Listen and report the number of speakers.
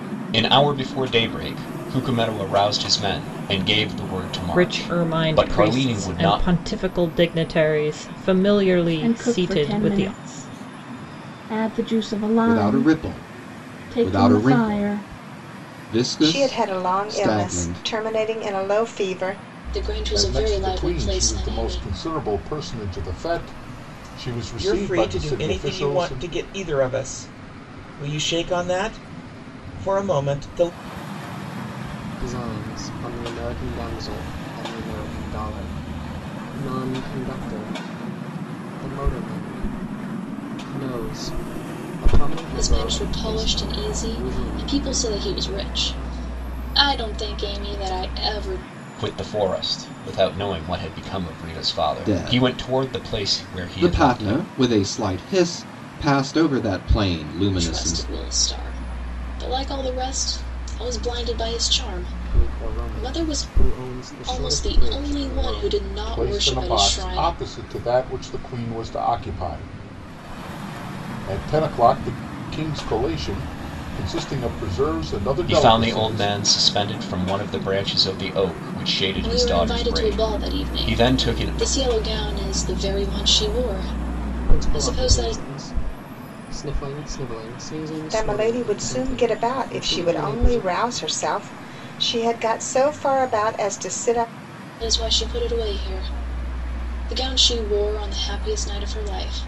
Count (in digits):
9